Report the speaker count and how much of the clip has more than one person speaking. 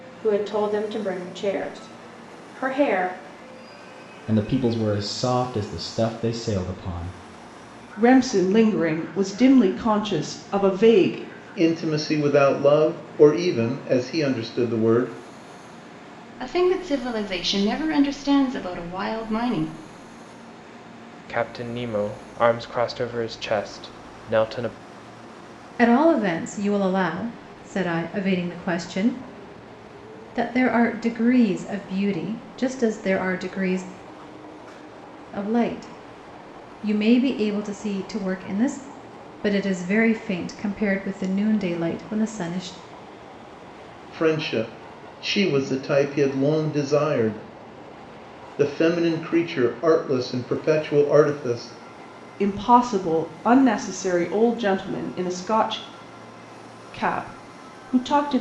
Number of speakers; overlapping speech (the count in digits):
7, no overlap